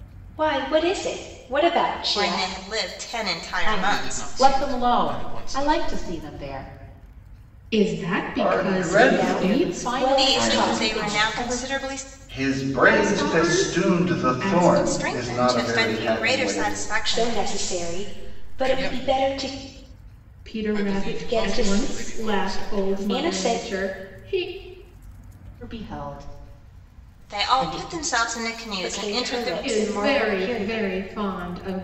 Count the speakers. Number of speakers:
6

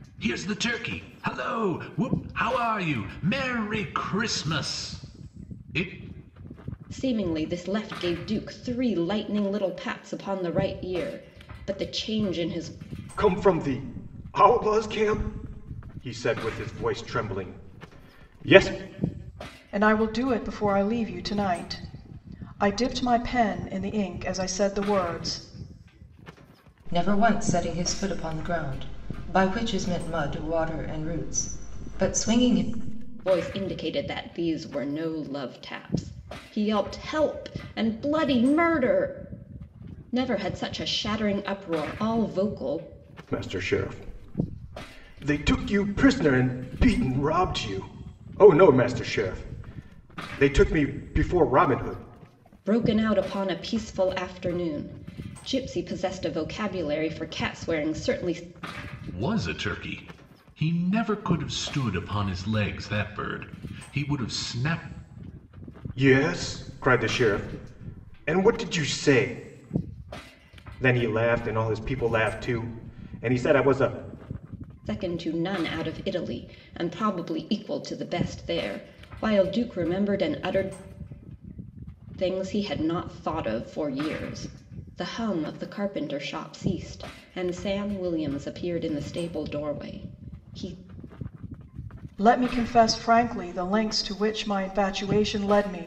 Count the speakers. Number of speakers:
5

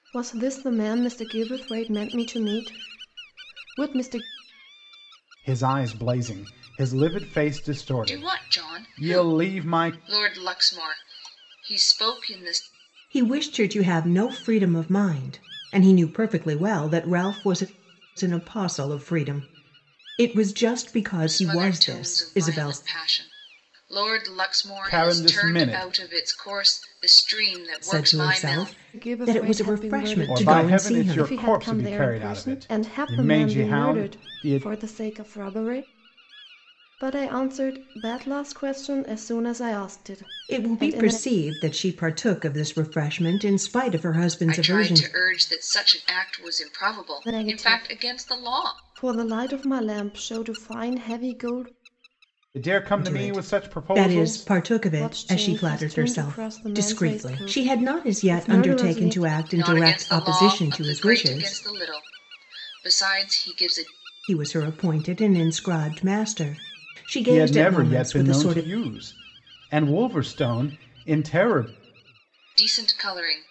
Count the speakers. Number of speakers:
4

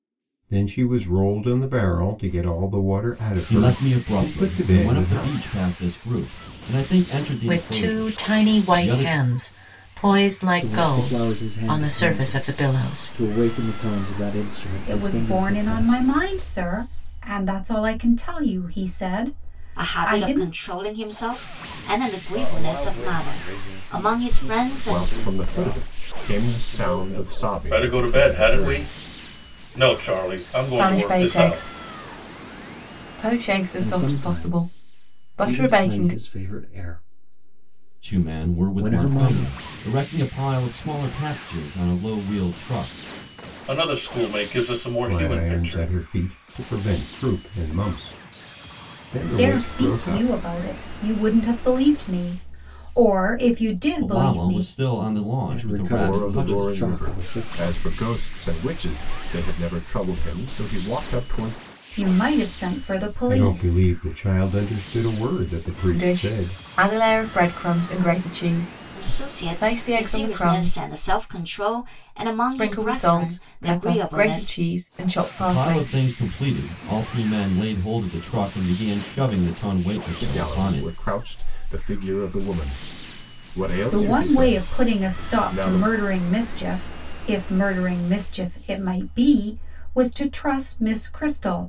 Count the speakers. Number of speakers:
10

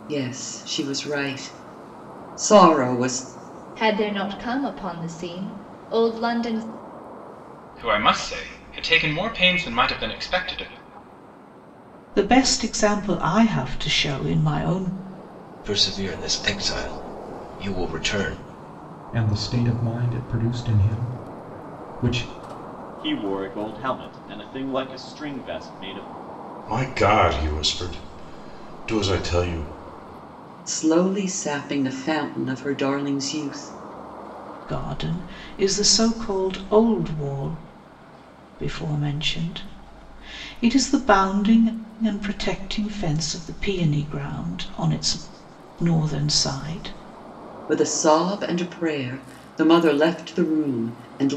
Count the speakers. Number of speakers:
8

